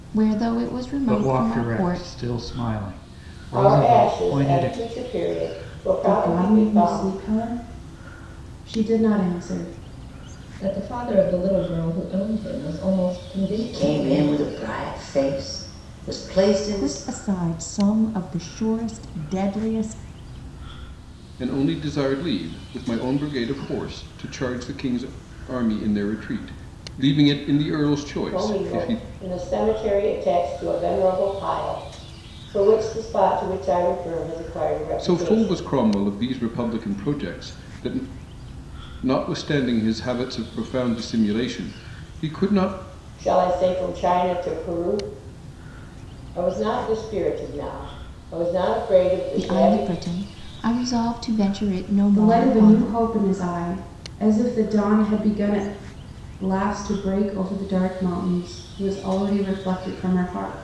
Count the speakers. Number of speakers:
8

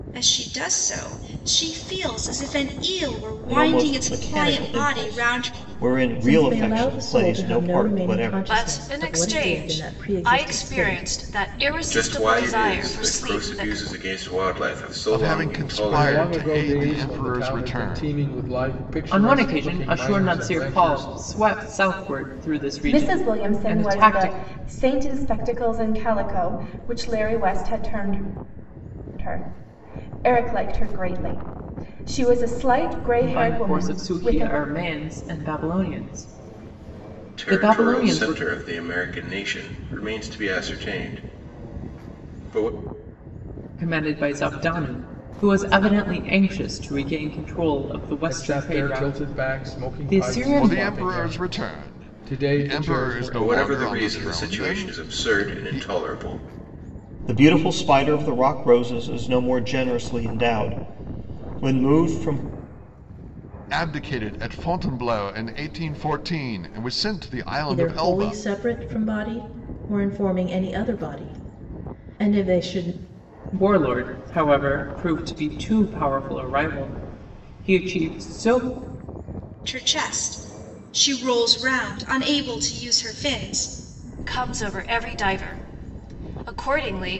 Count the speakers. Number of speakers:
9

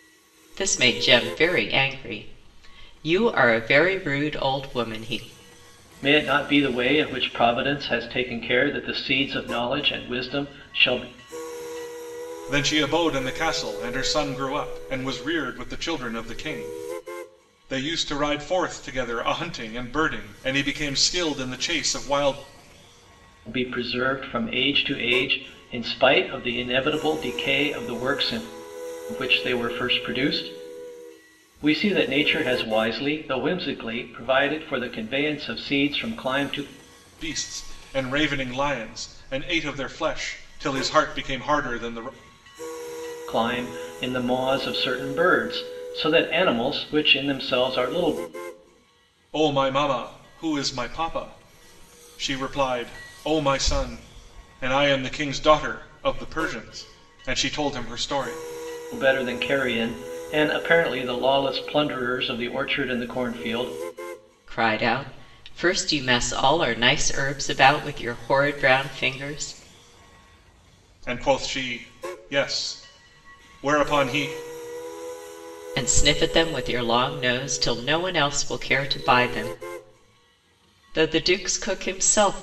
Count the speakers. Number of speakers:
3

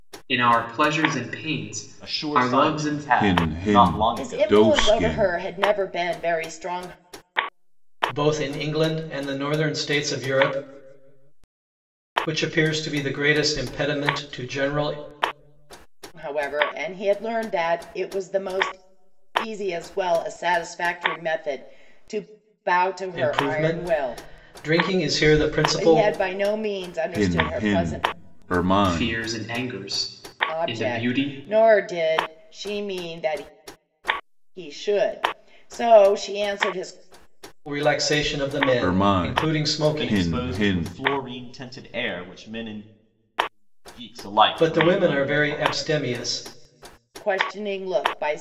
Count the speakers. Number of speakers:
5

